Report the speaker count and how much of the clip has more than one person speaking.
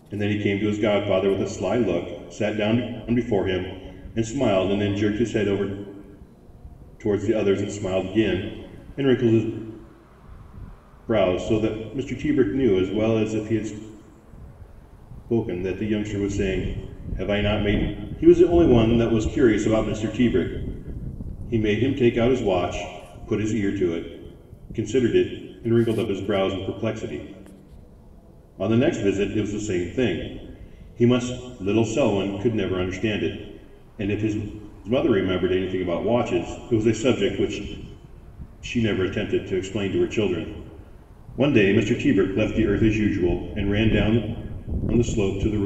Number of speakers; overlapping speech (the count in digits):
1, no overlap